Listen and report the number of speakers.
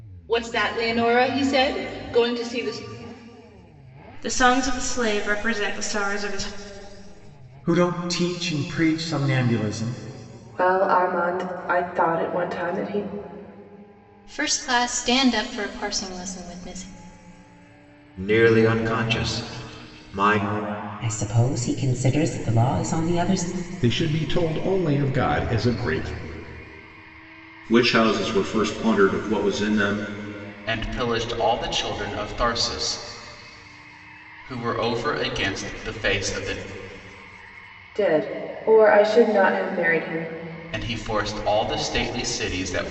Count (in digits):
10